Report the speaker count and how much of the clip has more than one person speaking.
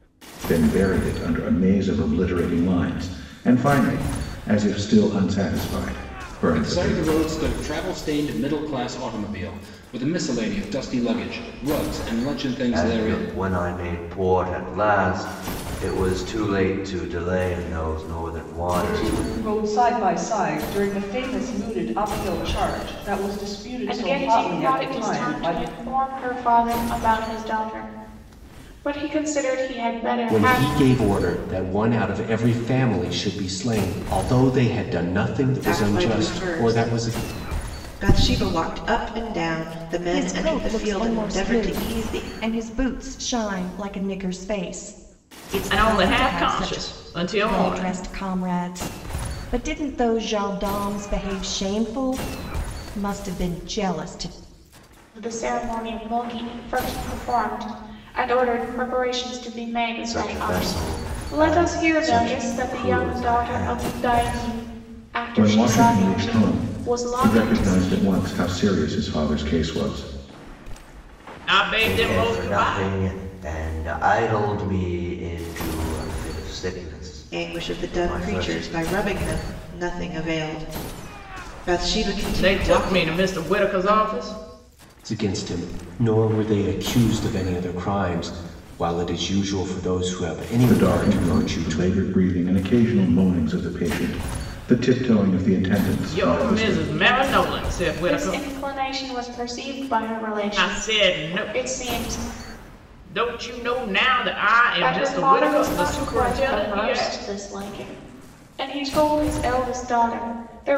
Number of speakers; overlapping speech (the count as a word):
nine, about 26%